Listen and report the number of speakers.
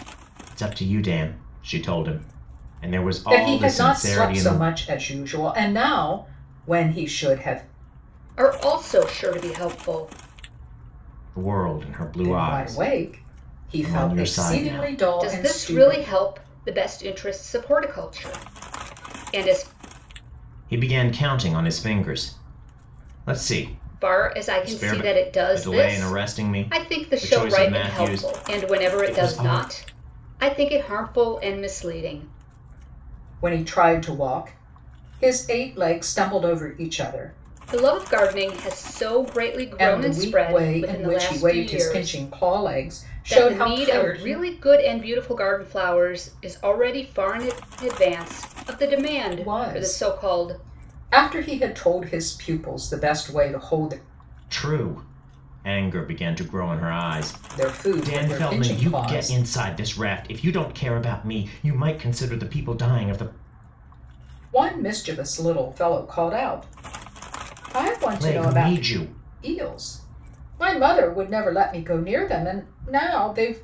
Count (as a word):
three